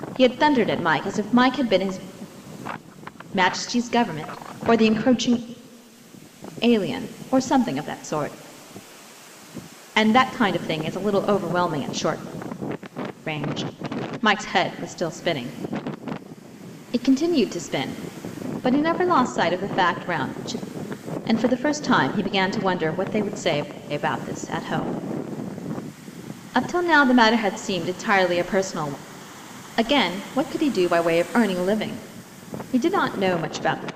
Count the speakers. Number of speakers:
one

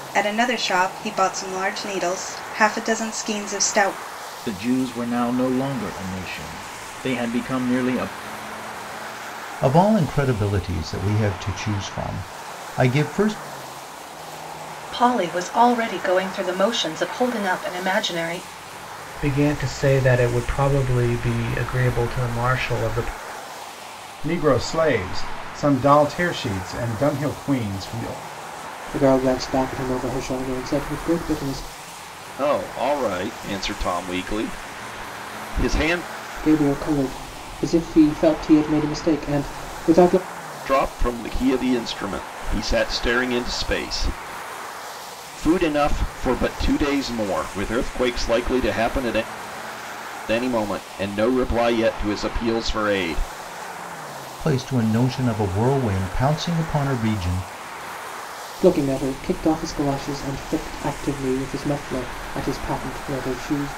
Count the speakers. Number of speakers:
eight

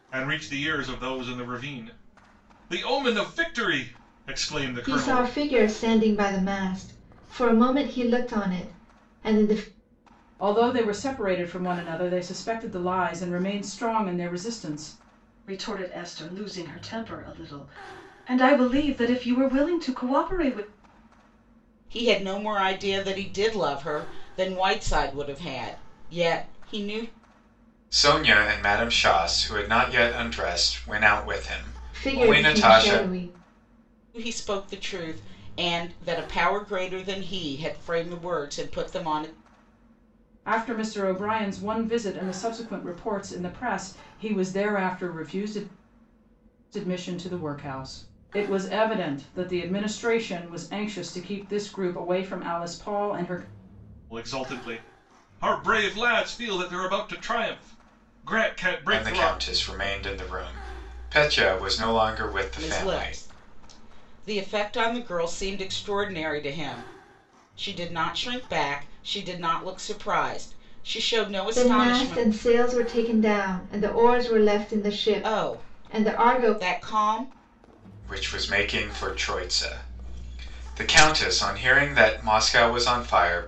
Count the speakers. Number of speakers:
six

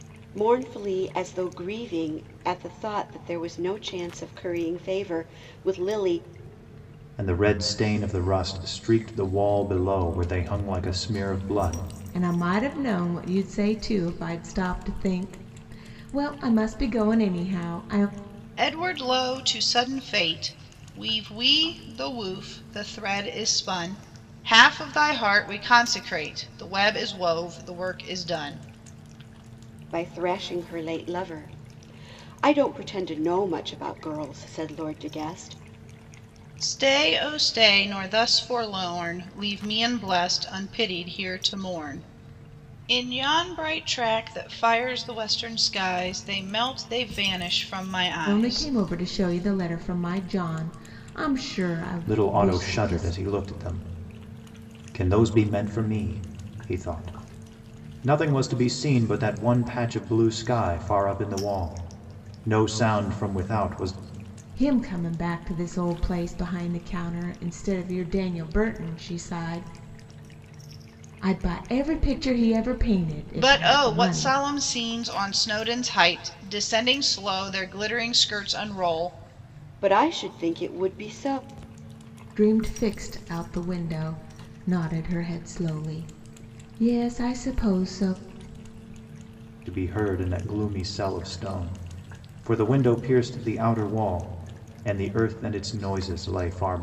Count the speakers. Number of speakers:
four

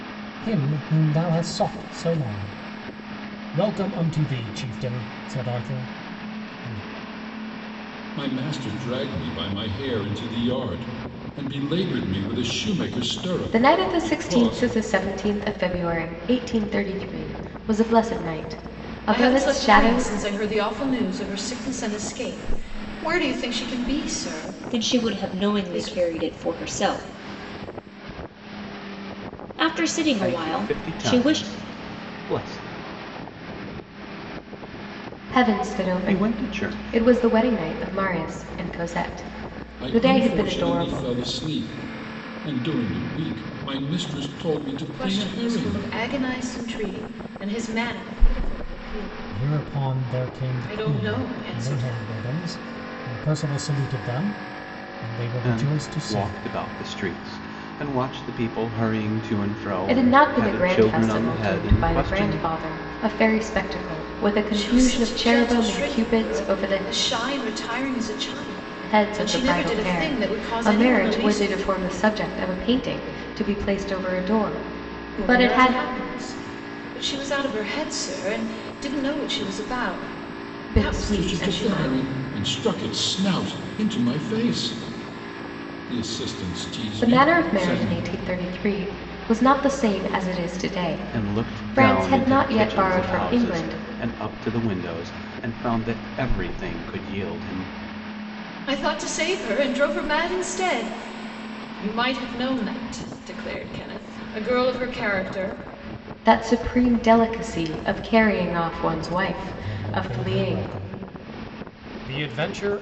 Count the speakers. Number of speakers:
six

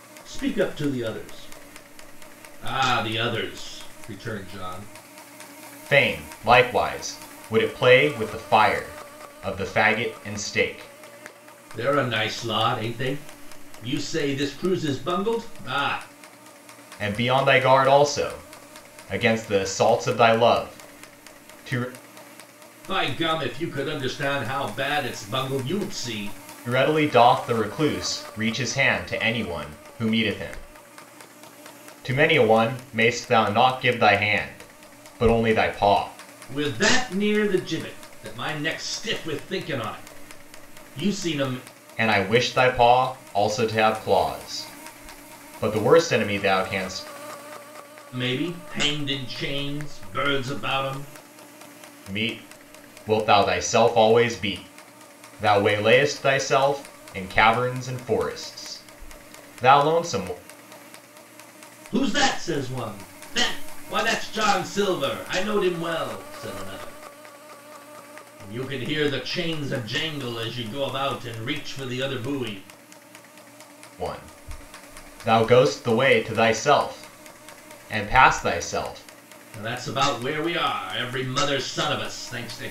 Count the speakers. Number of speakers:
two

